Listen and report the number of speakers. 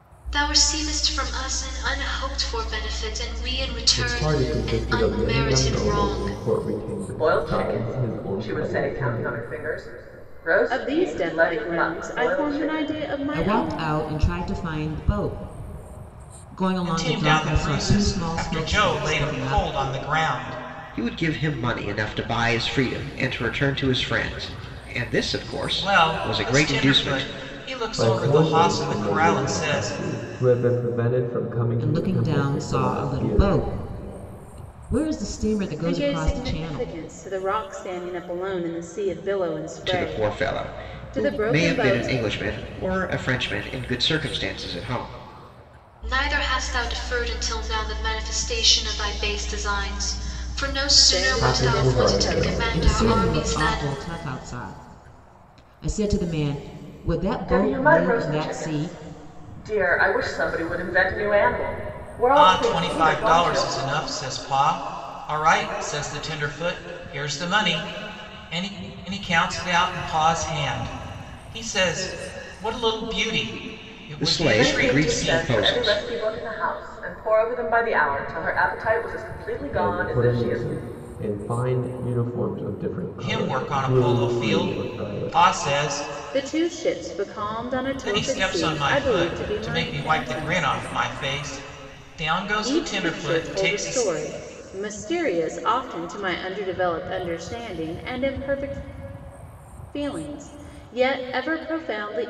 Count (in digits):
7